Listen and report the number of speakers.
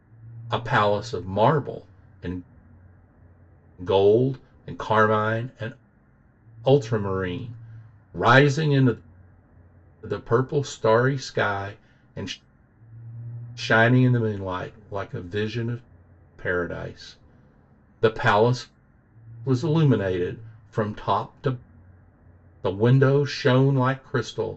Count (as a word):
one